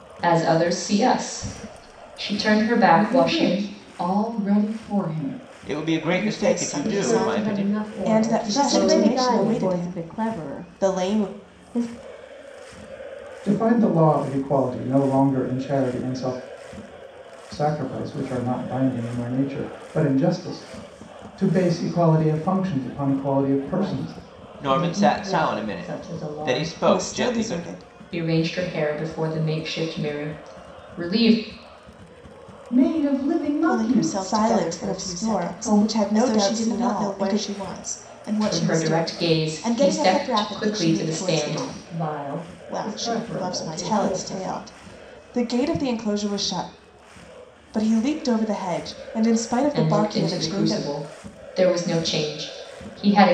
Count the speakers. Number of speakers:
eight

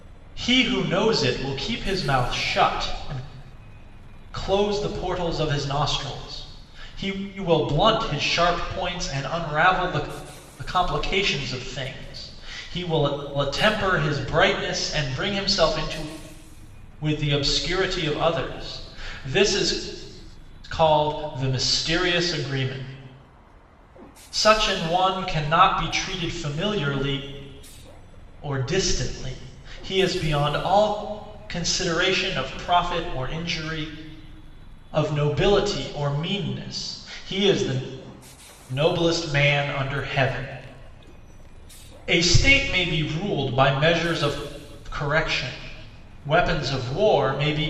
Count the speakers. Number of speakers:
one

